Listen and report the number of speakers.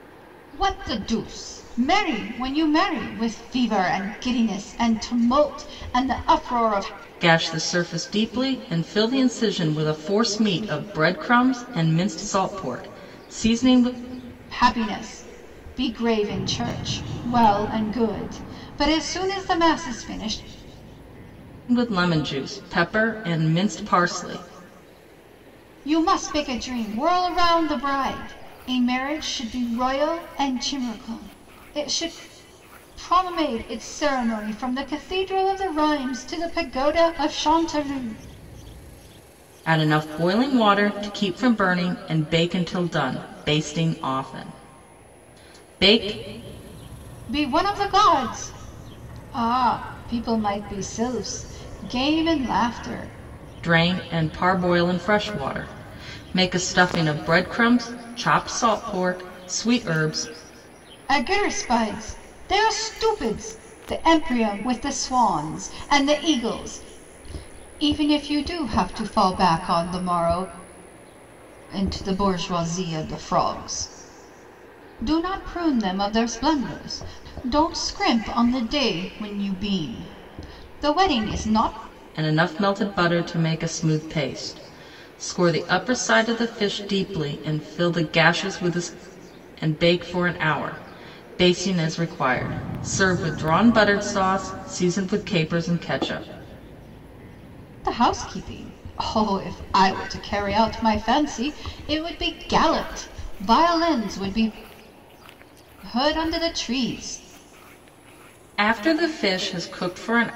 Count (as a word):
two